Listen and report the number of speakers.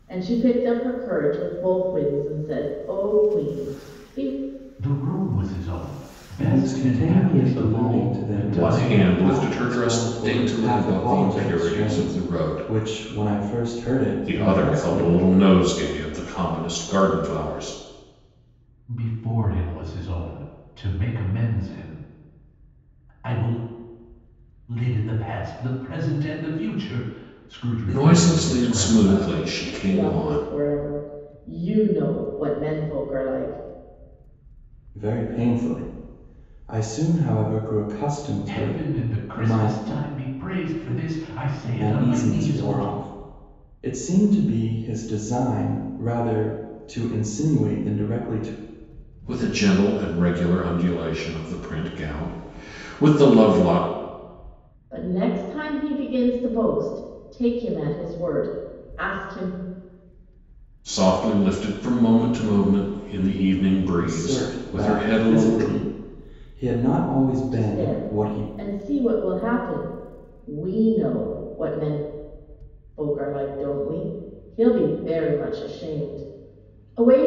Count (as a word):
four